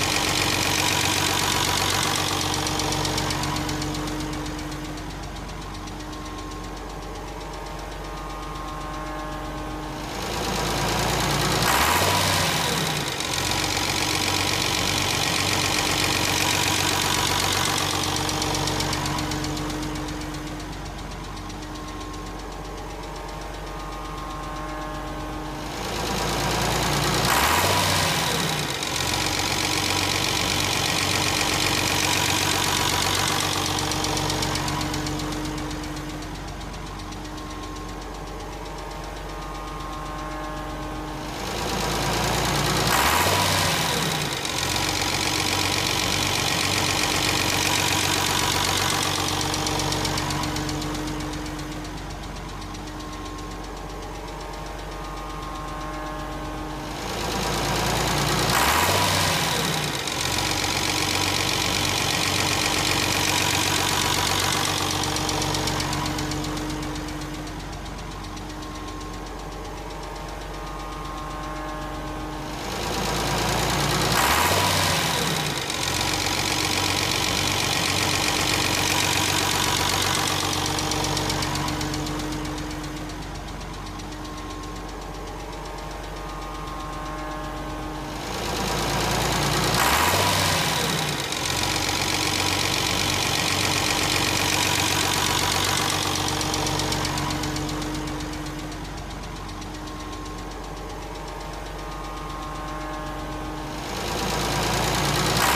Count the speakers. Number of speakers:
0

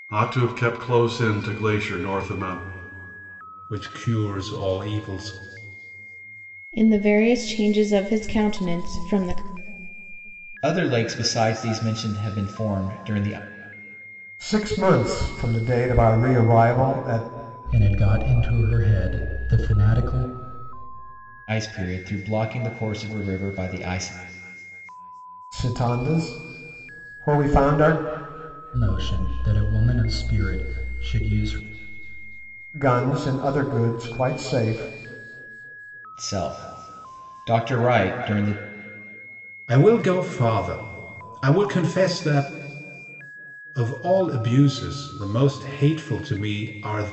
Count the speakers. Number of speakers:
6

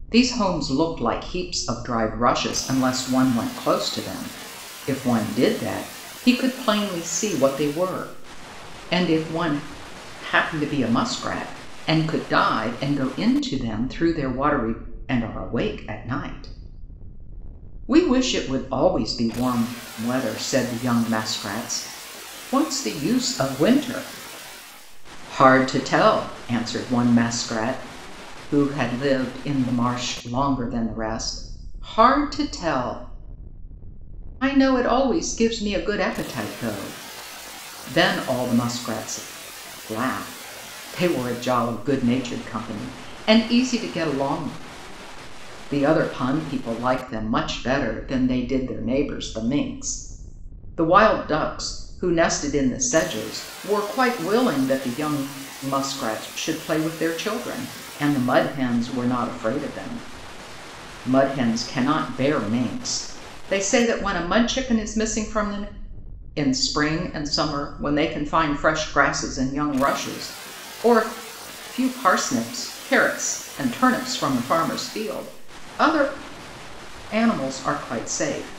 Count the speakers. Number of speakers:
1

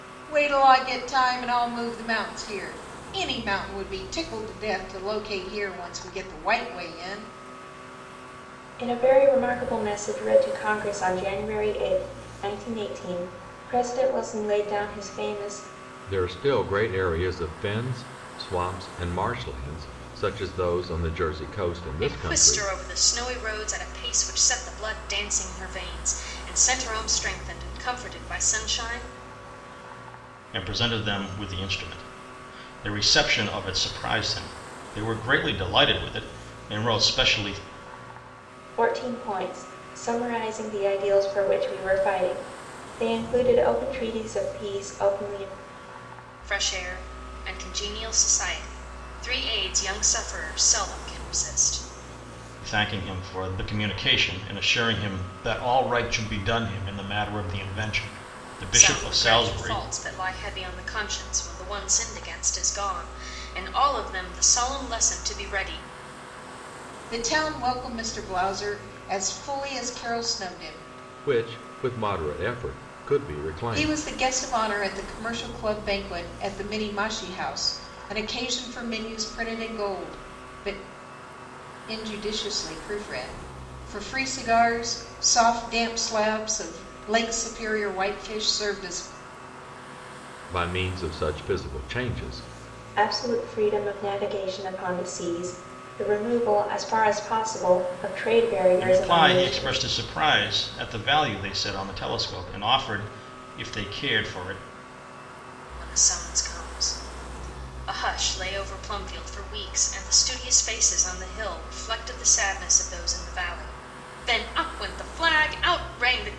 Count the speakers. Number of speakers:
5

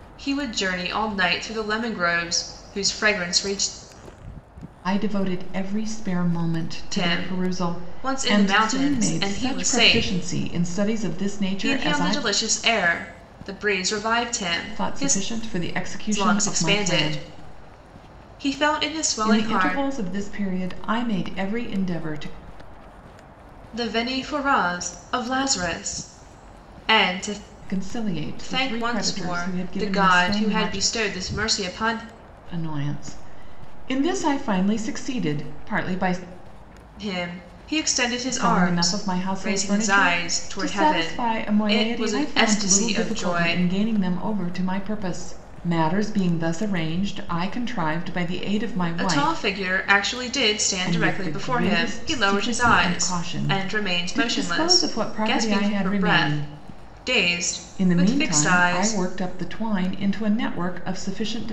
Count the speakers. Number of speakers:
2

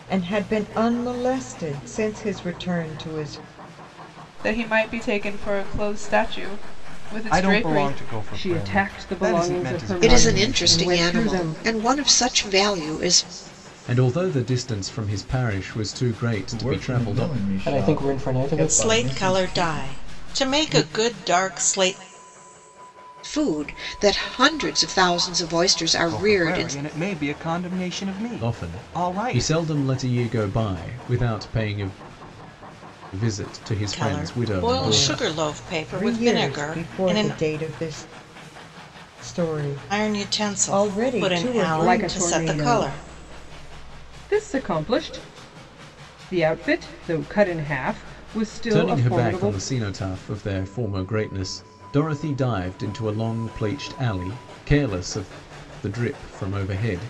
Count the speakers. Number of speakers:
9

